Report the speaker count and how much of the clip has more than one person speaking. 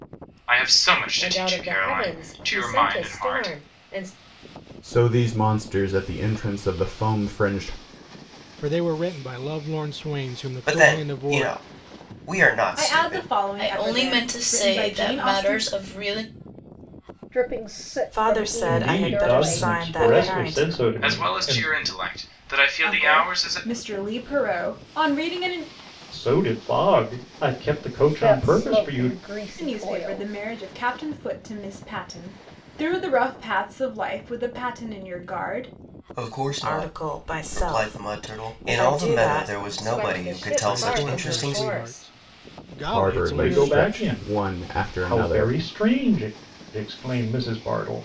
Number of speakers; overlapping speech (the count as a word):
ten, about 42%